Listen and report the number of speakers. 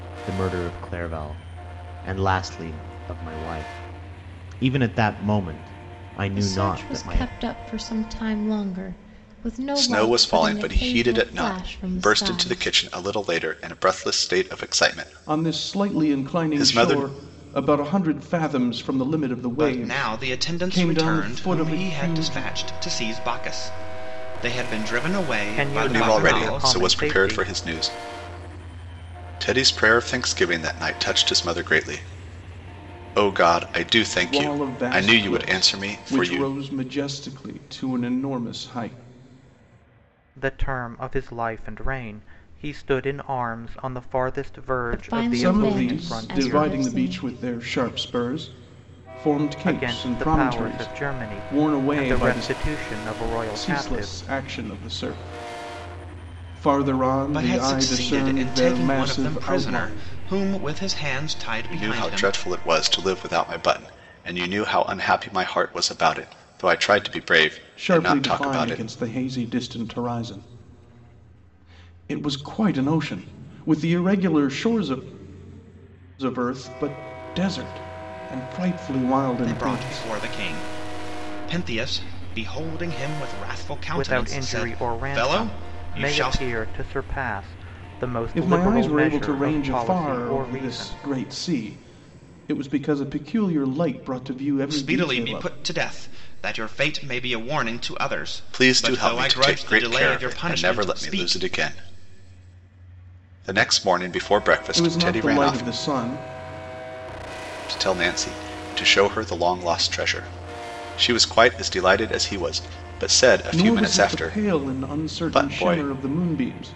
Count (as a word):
six